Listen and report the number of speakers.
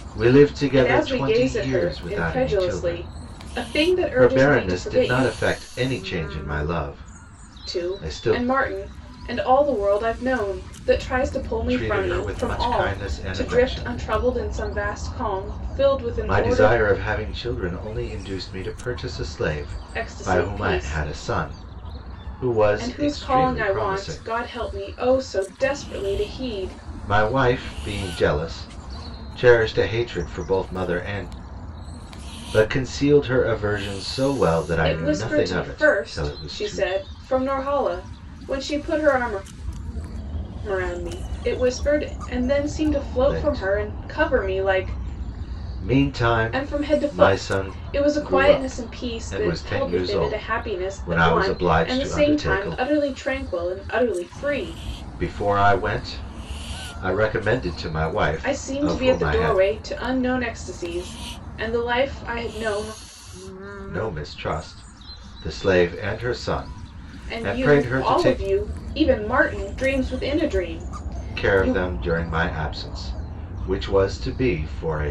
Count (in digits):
2